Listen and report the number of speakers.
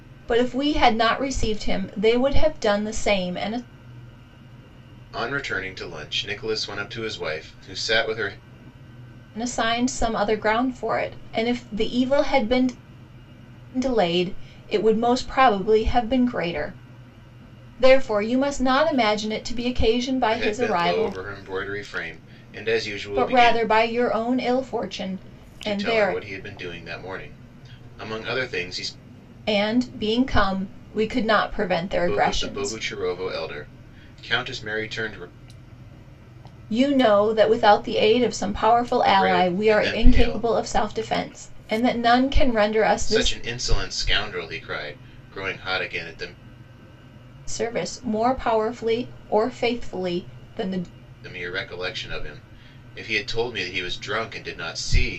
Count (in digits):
2